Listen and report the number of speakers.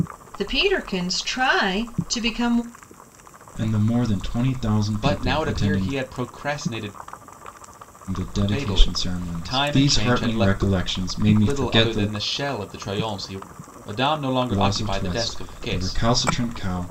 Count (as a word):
three